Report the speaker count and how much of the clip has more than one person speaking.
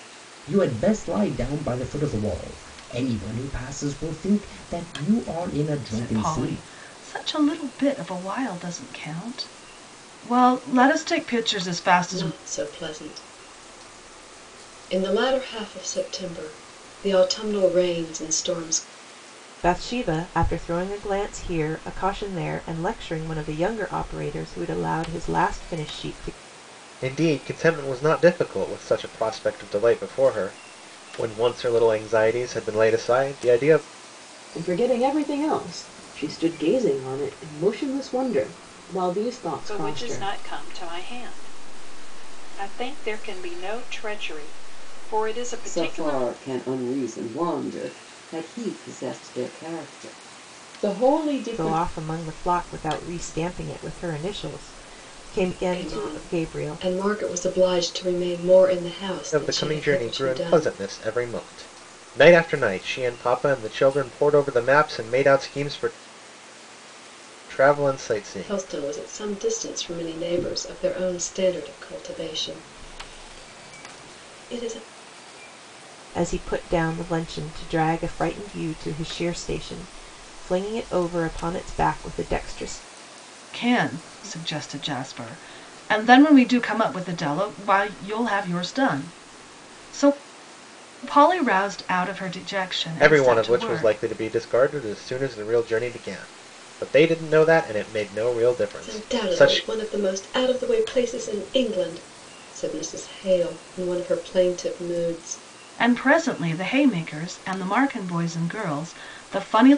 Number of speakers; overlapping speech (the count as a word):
eight, about 7%